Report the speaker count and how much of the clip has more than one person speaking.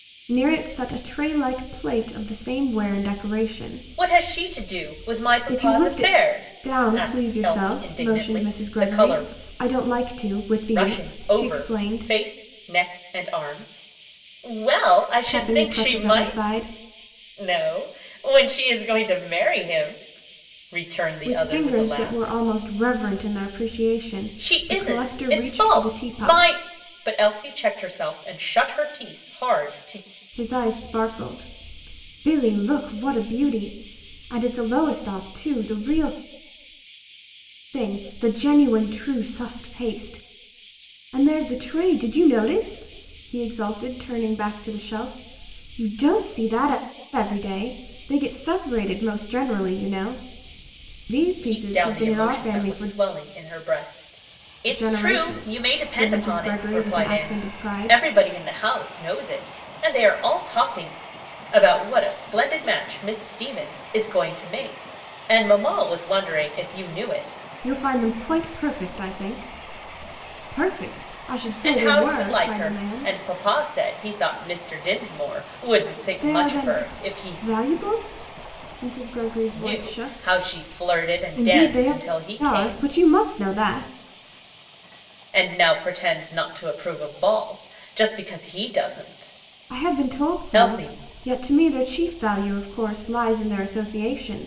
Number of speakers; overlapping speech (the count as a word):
two, about 24%